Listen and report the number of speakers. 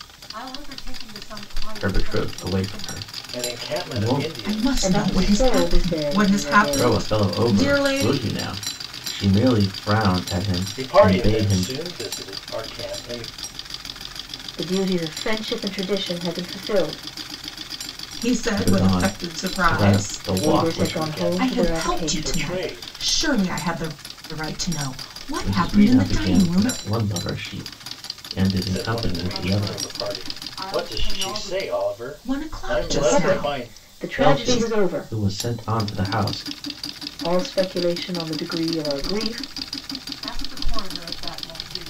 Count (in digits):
5